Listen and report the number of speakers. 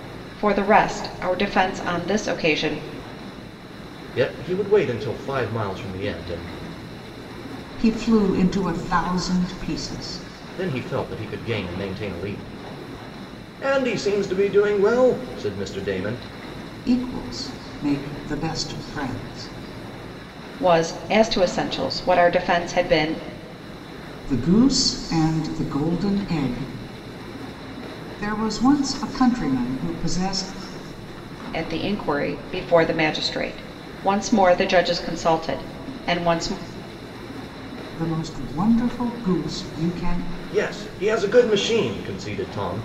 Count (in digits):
3